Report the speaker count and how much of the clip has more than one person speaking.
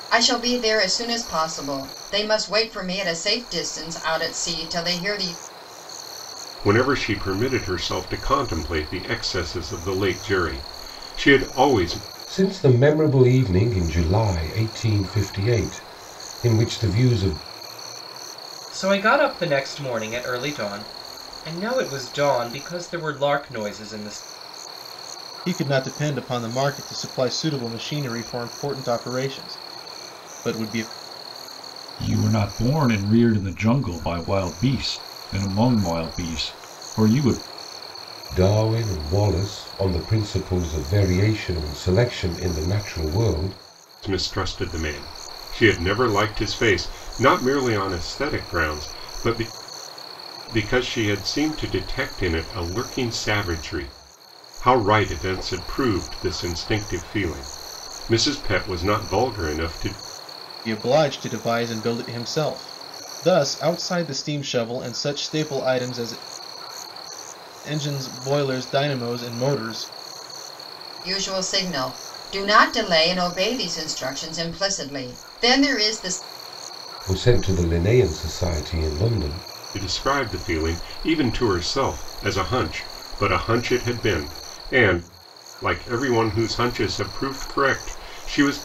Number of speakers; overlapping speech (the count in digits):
6, no overlap